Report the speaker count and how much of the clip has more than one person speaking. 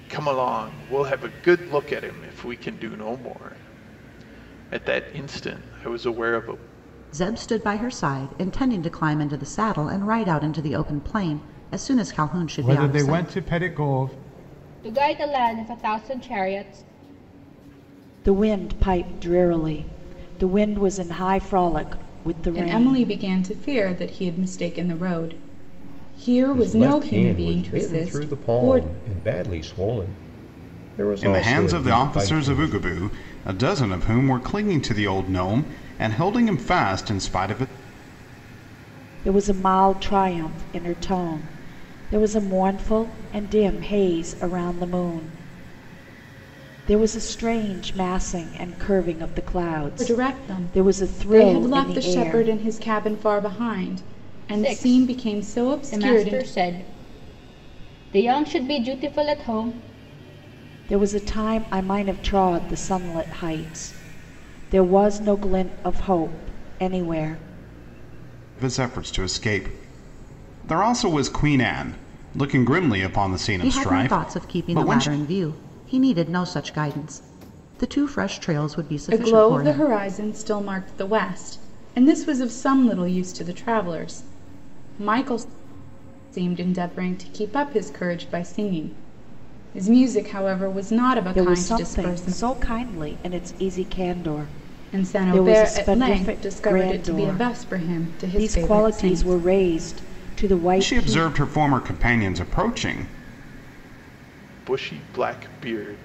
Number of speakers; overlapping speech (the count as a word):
seven, about 17%